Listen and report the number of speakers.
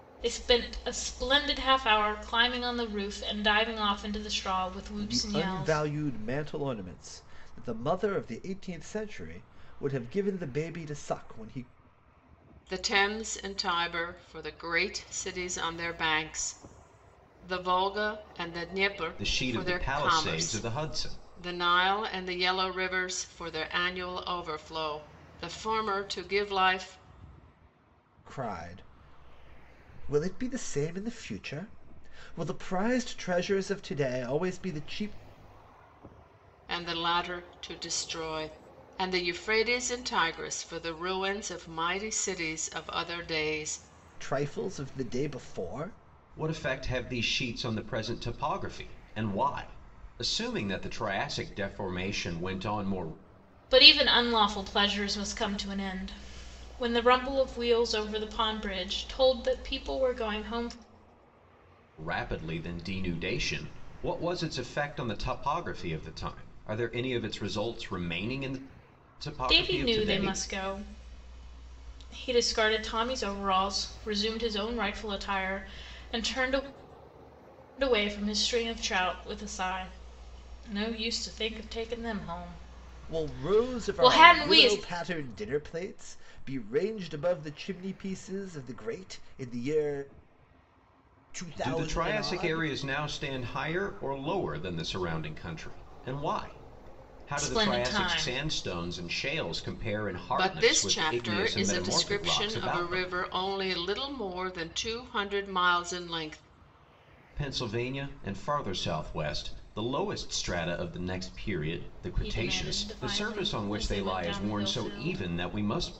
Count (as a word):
four